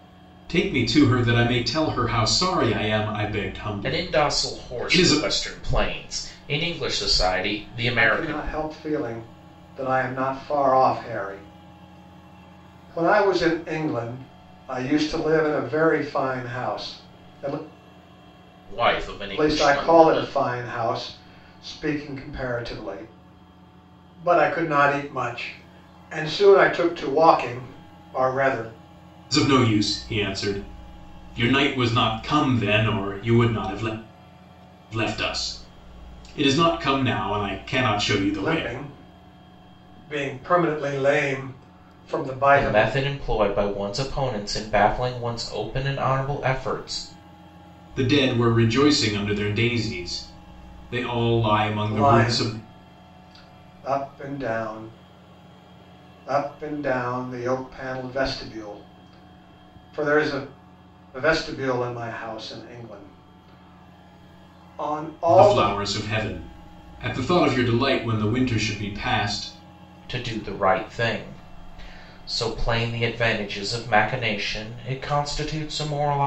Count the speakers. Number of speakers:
three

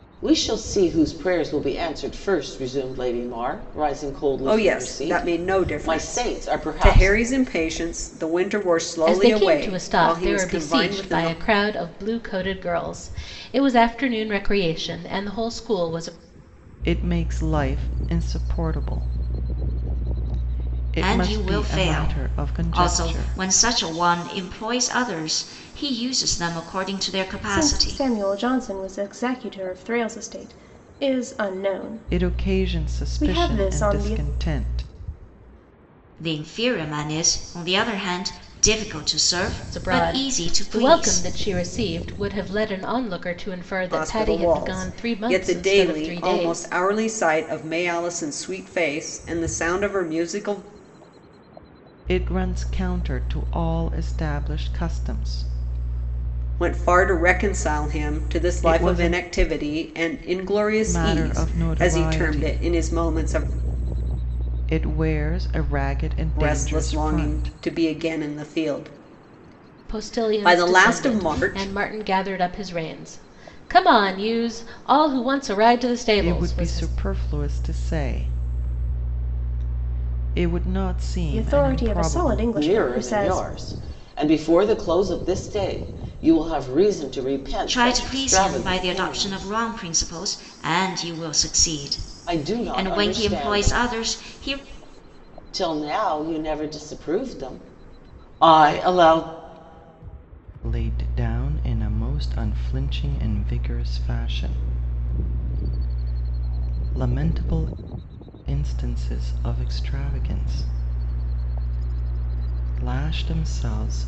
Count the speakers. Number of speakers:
six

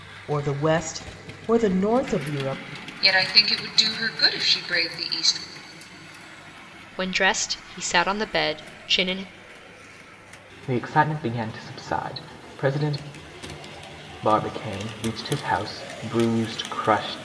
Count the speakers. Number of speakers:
four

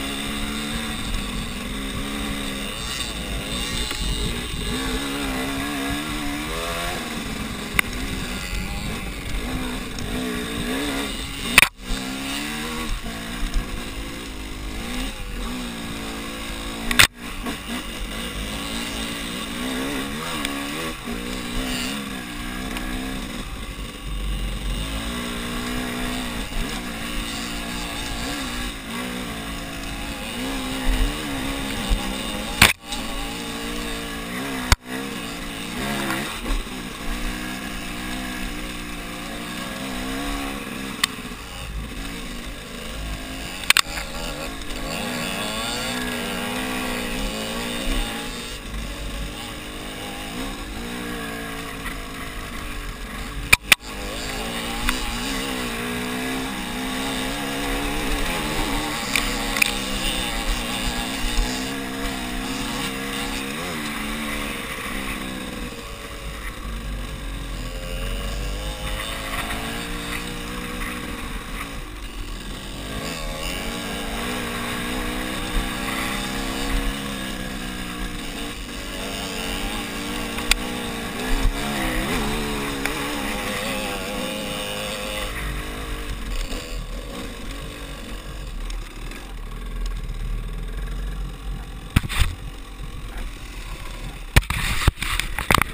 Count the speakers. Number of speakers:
zero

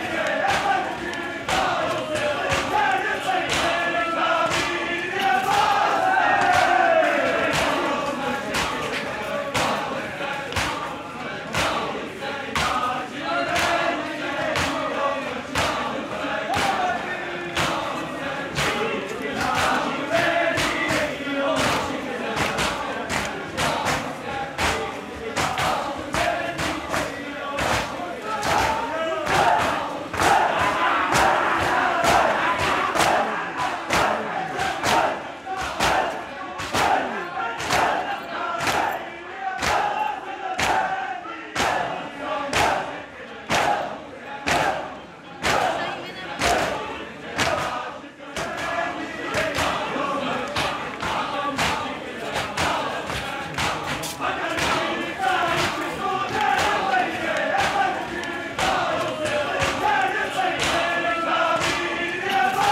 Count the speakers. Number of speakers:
zero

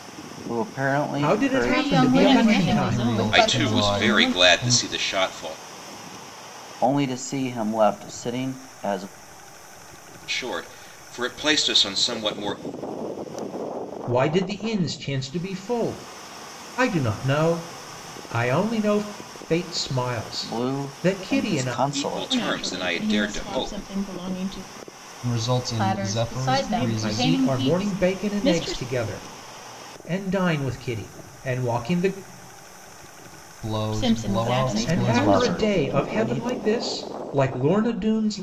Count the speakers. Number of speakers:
six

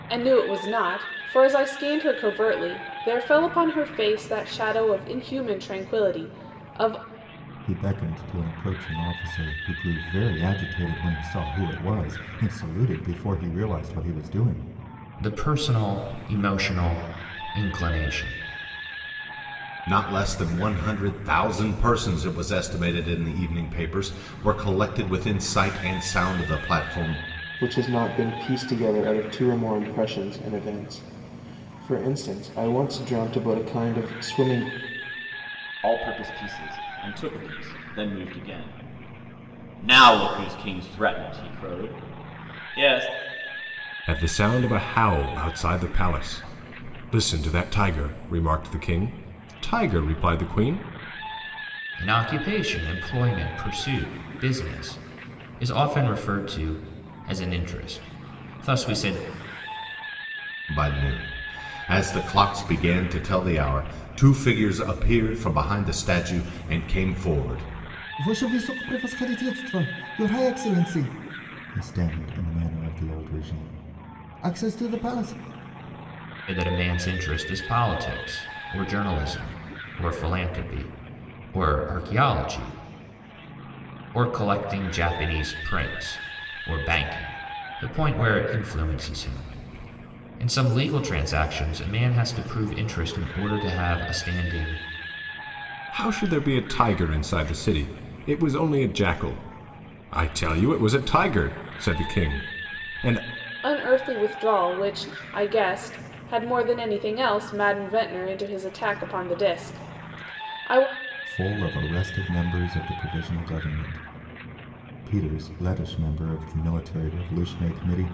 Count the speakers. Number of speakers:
seven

